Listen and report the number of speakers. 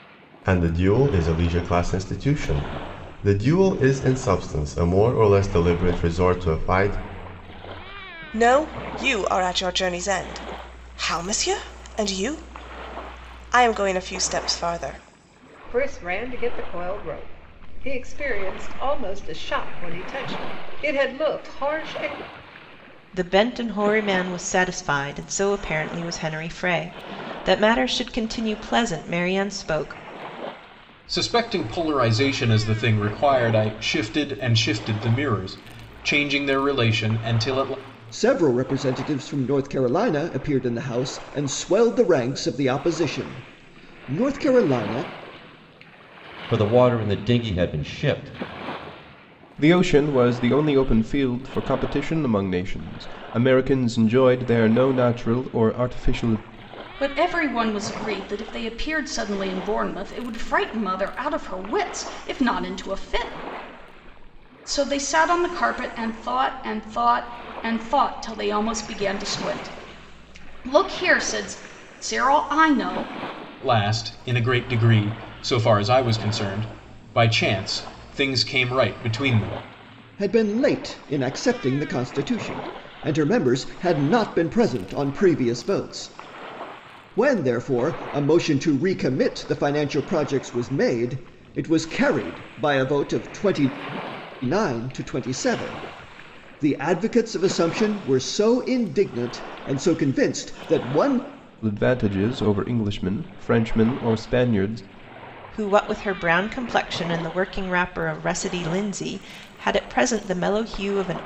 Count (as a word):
nine